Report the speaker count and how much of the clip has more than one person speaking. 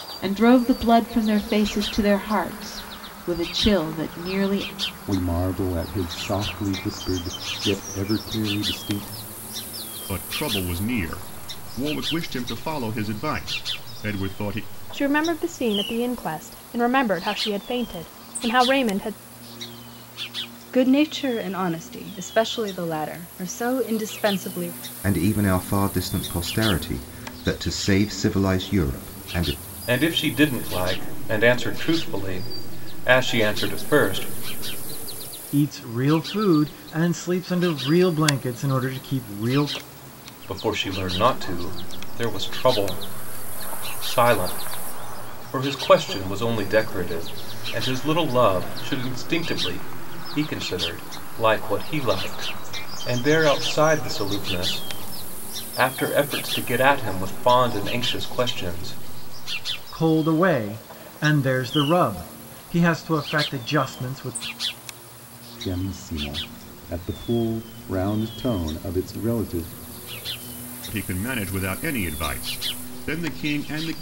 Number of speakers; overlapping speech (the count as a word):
eight, no overlap